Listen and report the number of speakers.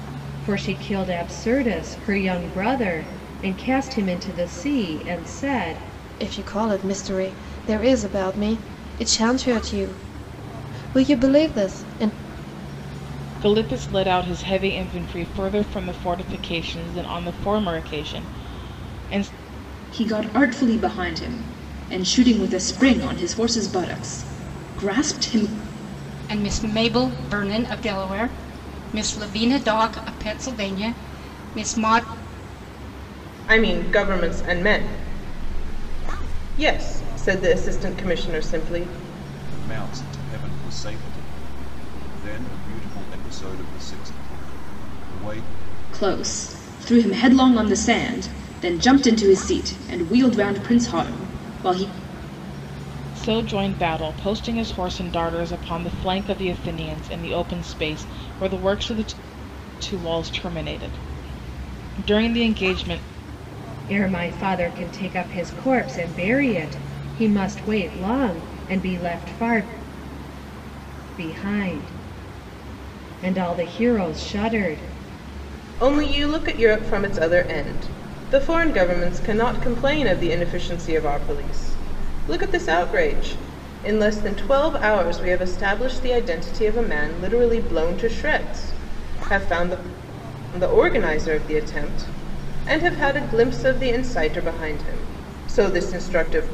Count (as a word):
seven